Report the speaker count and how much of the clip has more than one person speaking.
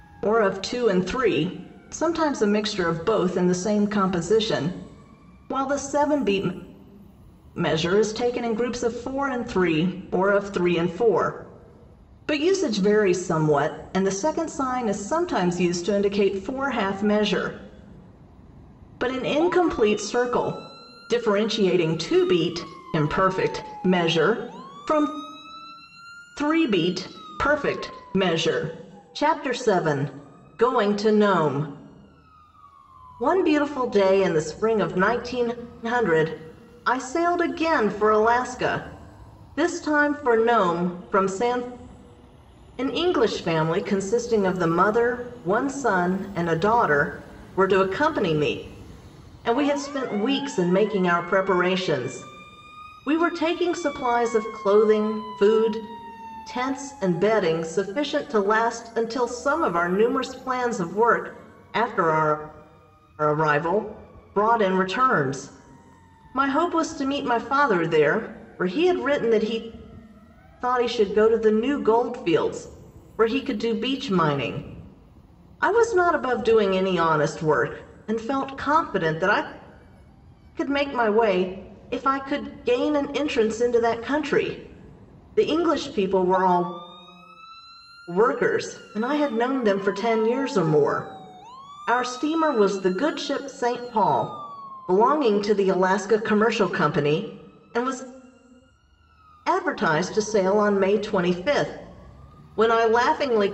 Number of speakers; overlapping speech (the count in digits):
1, no overlap